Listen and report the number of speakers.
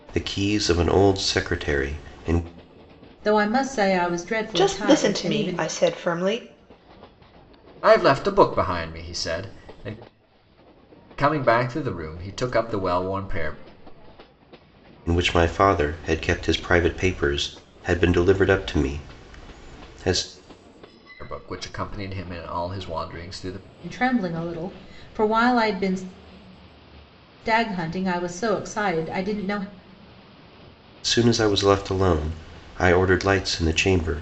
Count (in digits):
4